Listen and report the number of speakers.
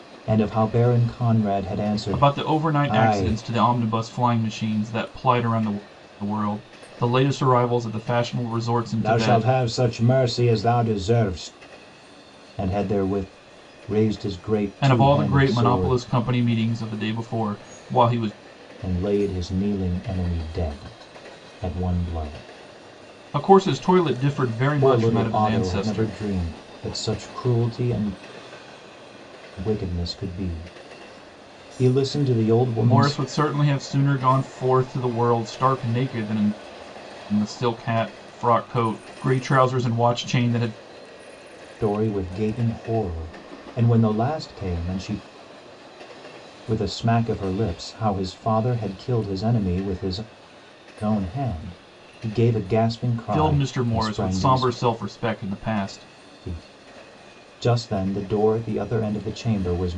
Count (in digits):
2